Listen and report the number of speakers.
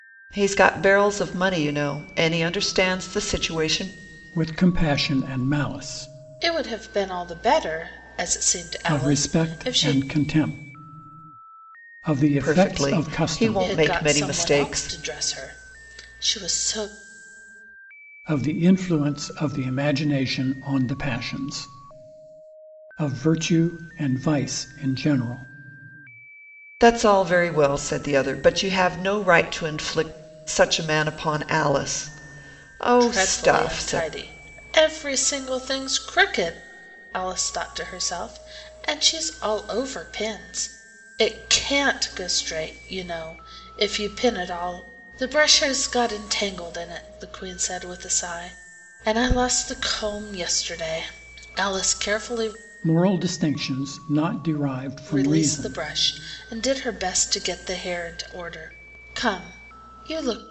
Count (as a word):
three